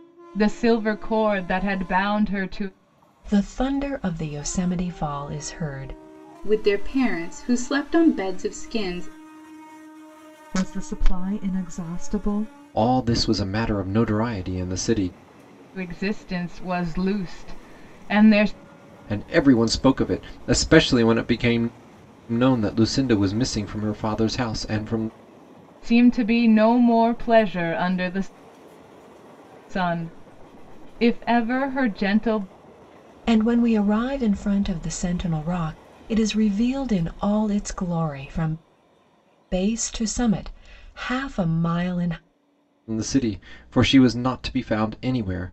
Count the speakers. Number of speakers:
five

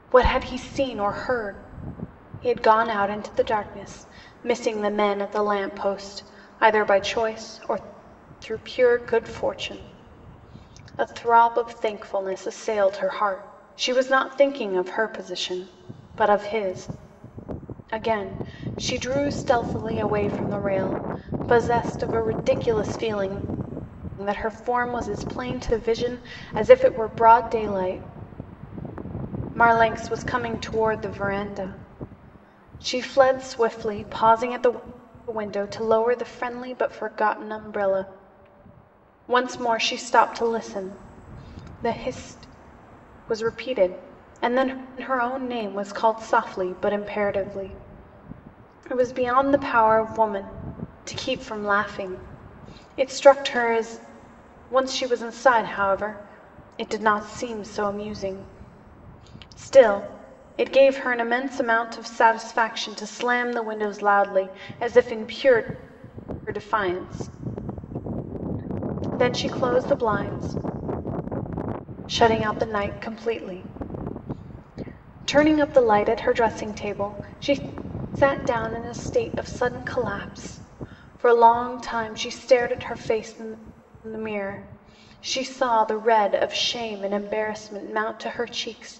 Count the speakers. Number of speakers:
one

